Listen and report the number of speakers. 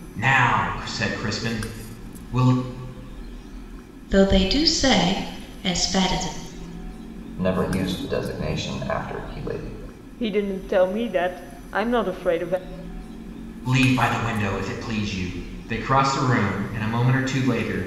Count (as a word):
four